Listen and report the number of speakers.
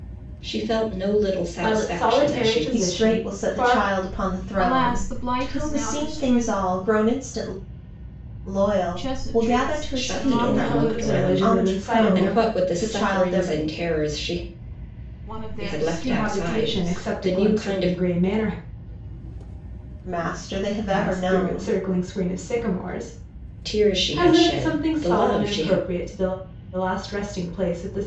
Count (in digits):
4